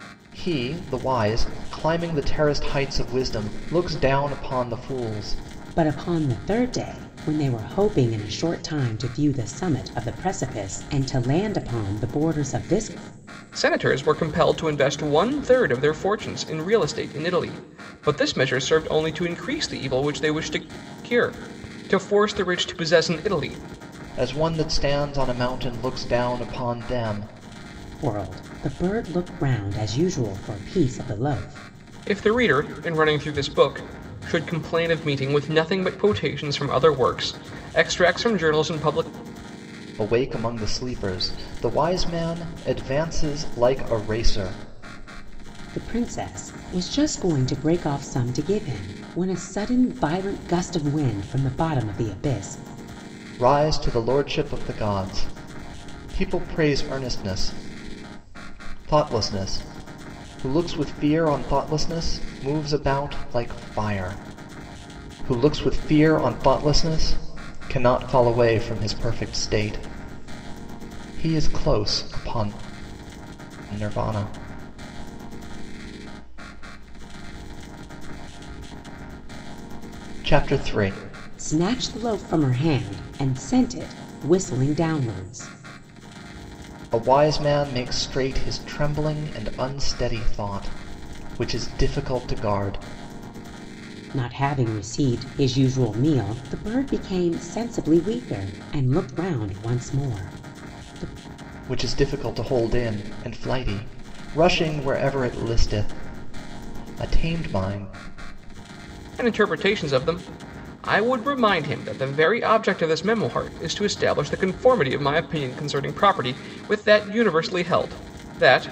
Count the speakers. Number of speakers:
3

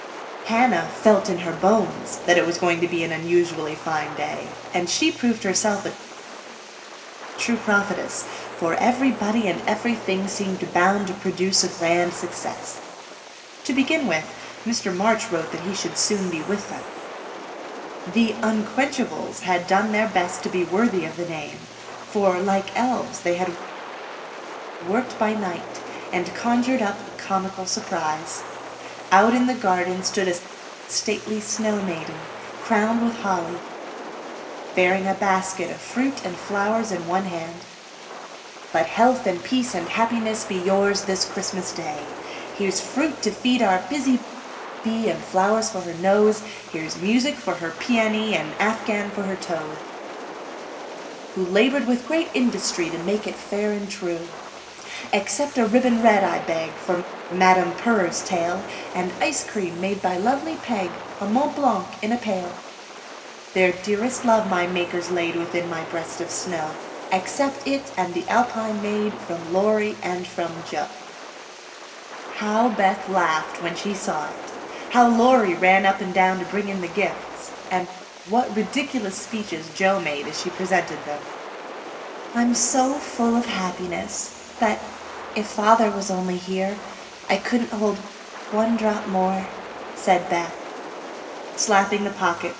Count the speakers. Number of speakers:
1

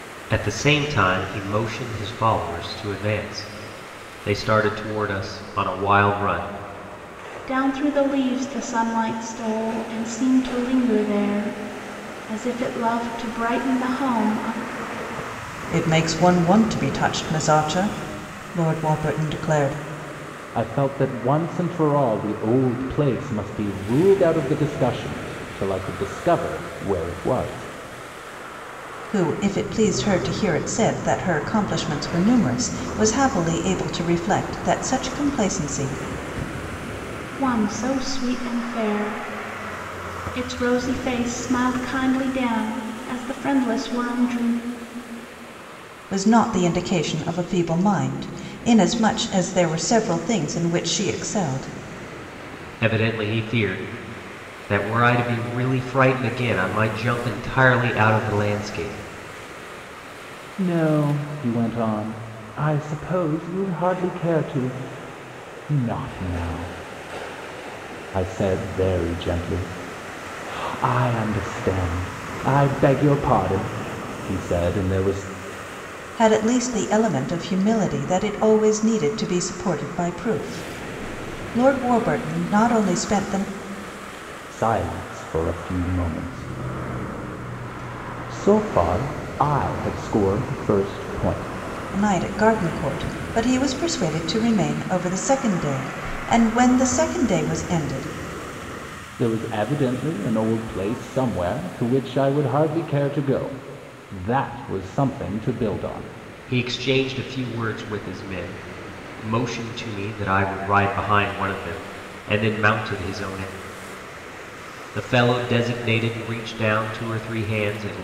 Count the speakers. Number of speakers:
4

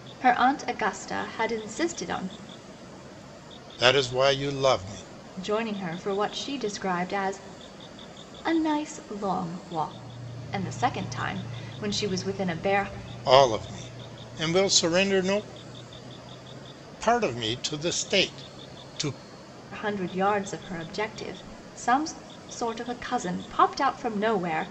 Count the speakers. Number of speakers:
2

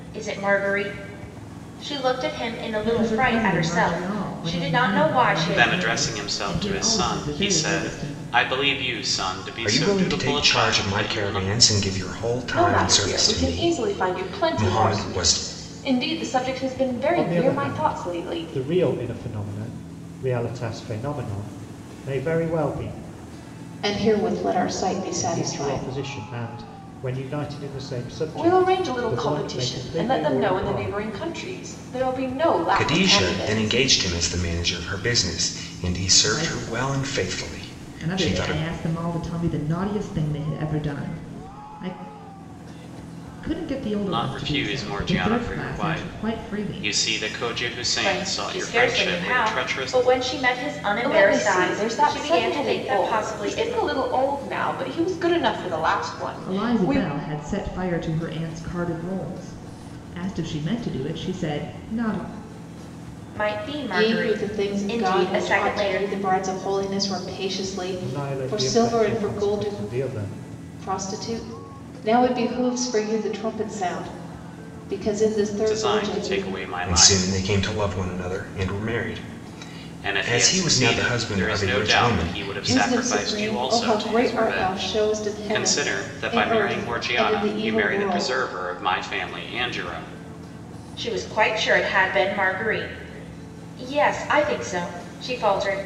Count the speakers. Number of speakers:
7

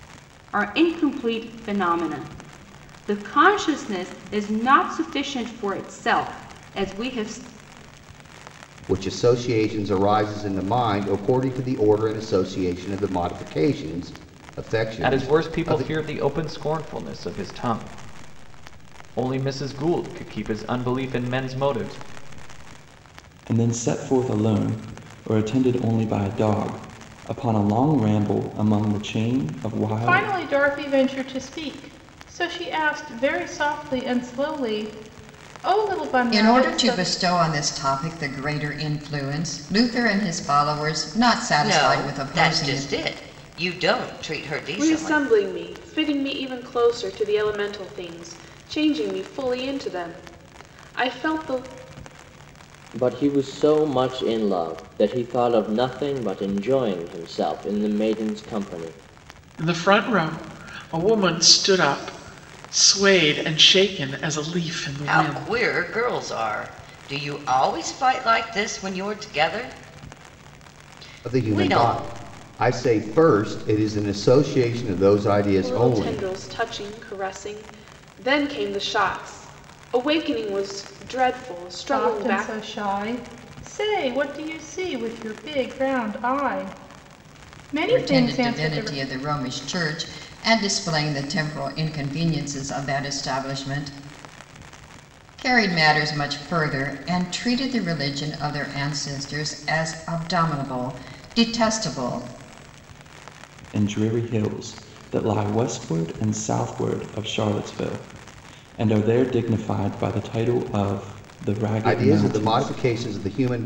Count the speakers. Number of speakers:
10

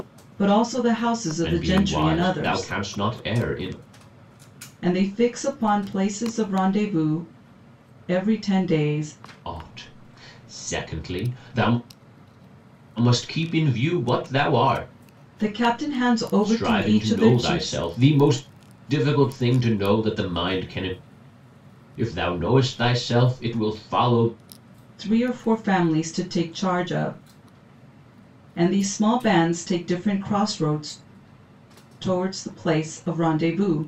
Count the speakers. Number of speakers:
2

